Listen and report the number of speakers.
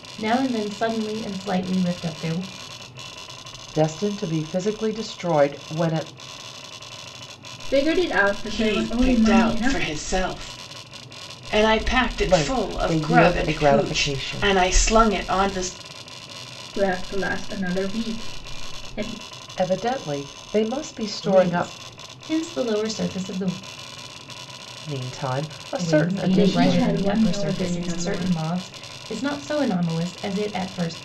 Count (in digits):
4